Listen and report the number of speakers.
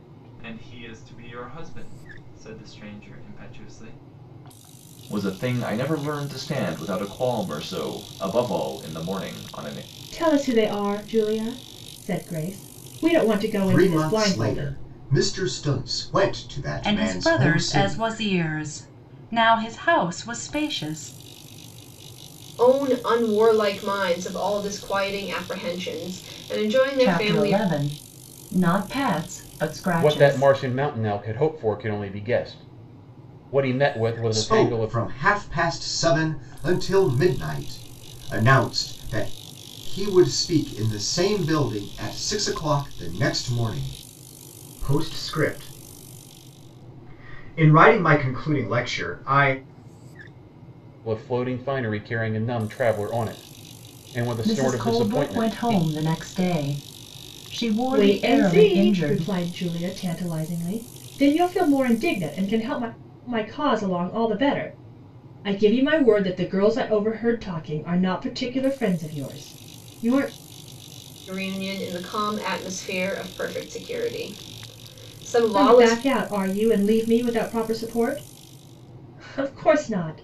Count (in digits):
8